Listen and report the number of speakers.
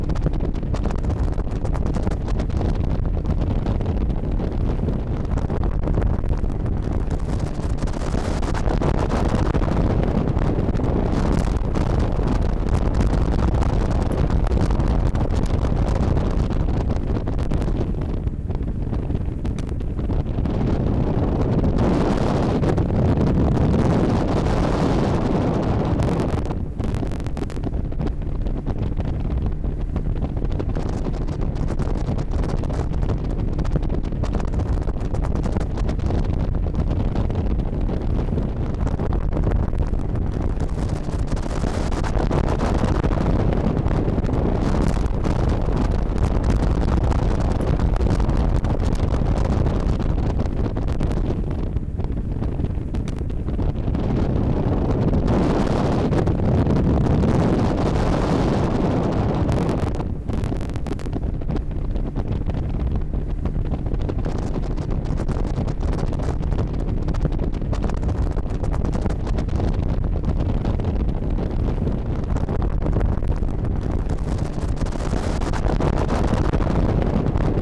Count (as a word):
zero